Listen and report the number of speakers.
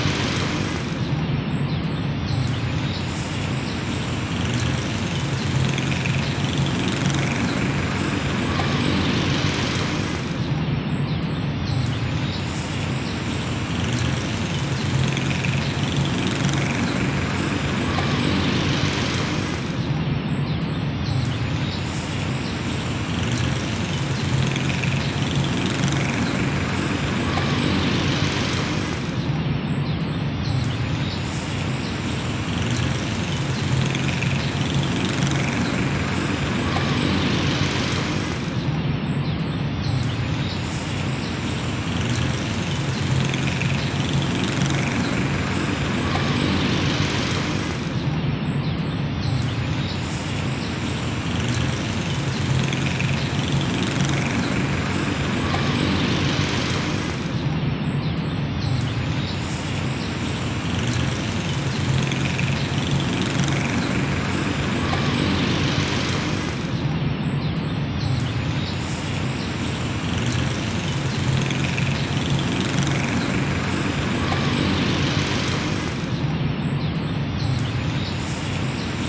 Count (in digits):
0